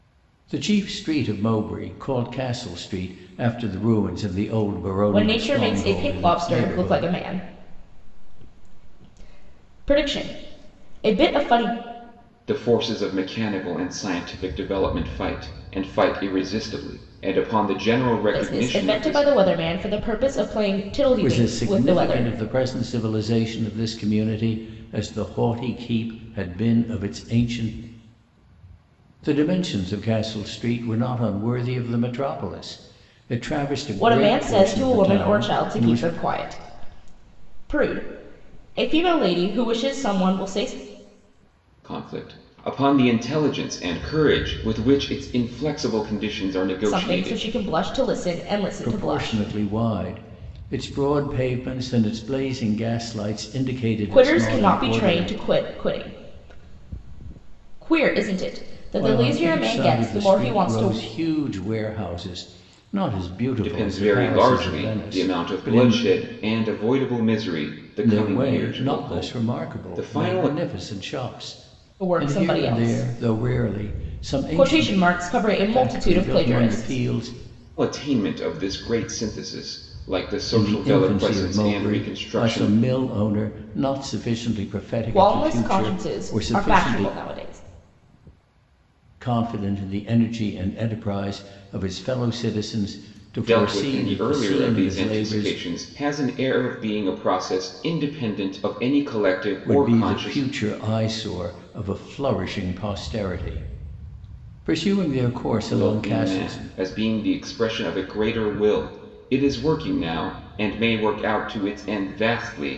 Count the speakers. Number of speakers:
three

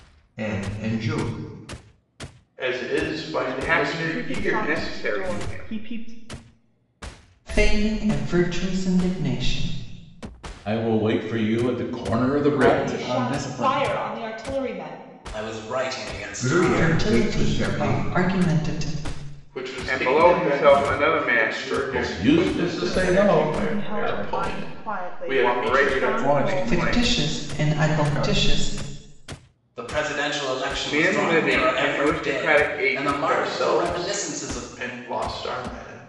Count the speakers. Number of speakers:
nine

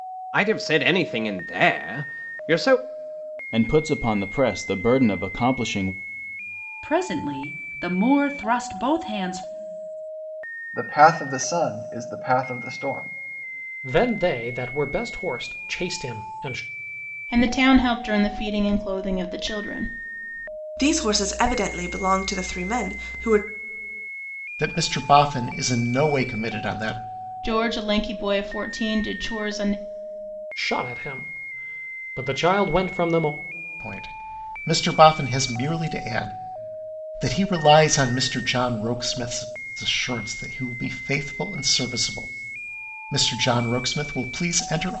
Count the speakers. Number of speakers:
eight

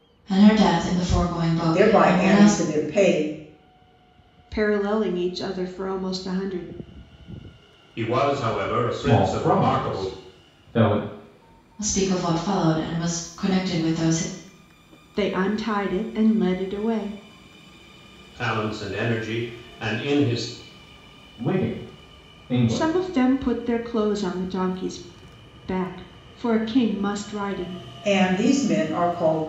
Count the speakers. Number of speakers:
five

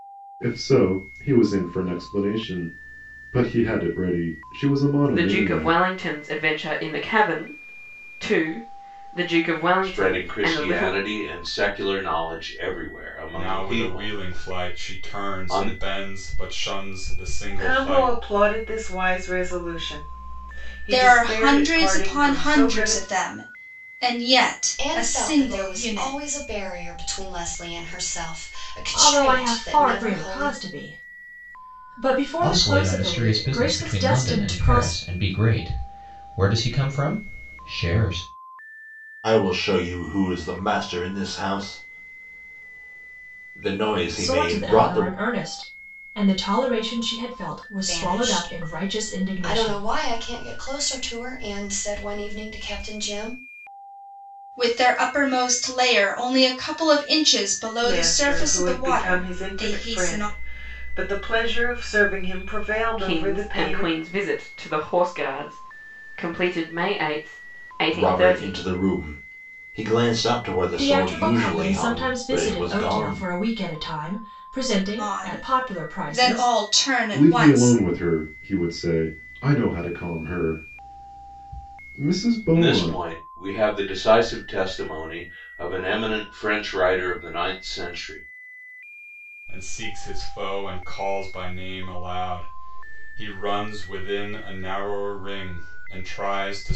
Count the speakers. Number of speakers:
ten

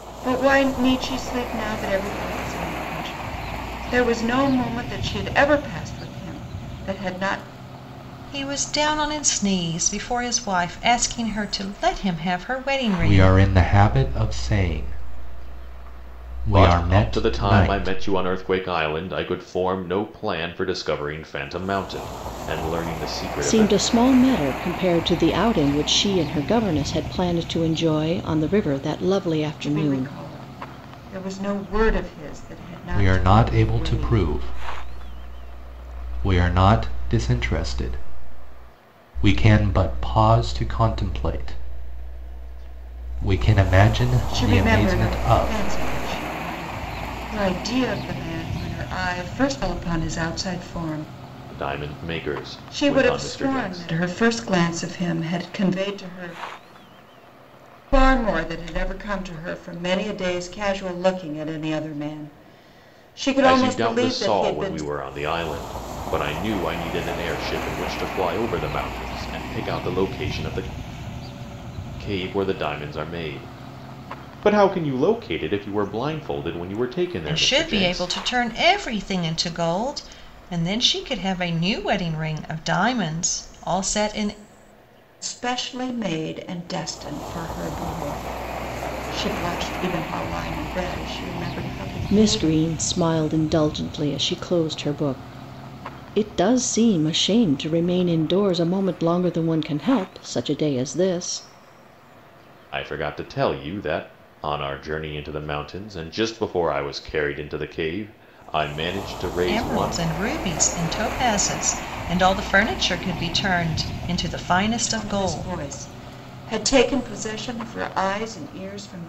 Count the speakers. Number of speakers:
five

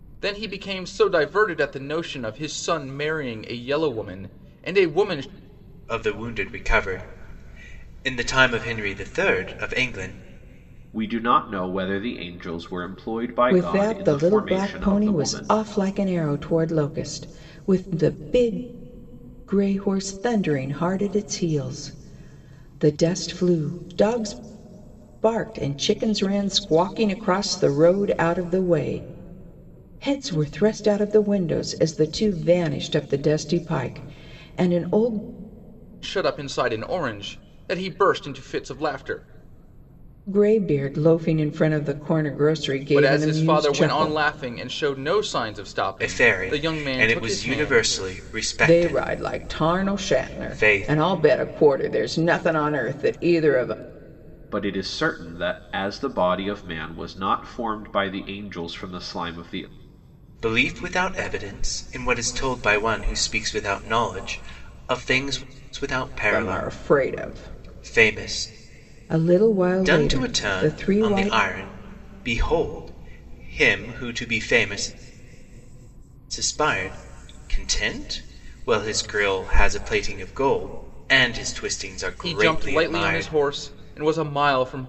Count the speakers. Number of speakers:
four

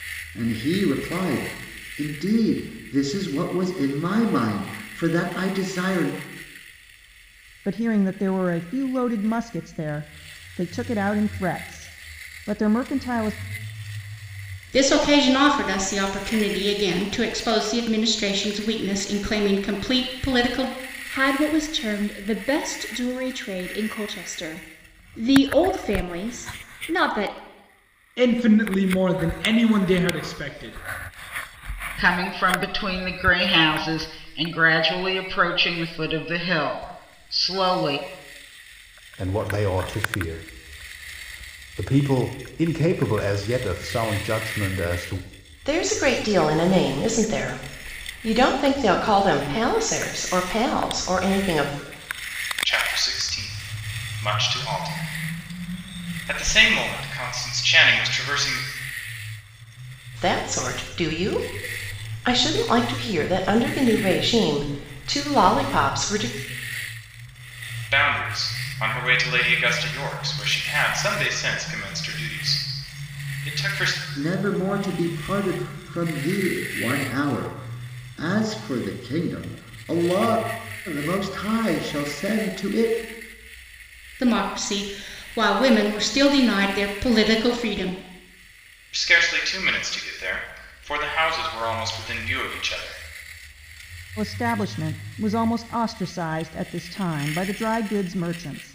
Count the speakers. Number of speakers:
nine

